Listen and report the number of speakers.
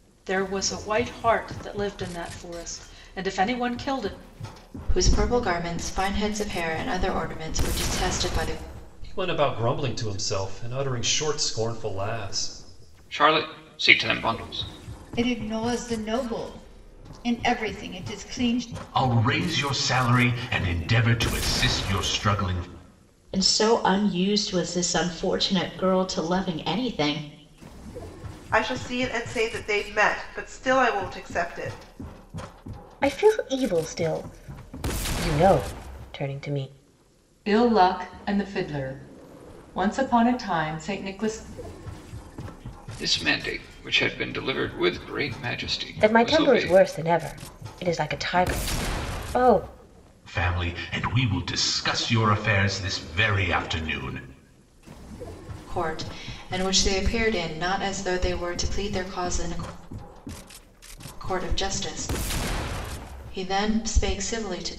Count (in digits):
10